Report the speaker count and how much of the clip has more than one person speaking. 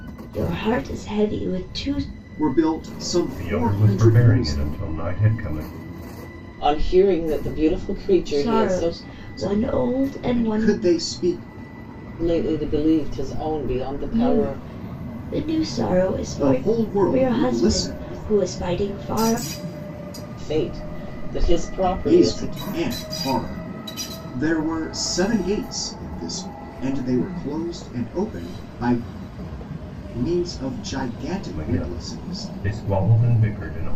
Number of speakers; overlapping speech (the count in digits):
4, about 21%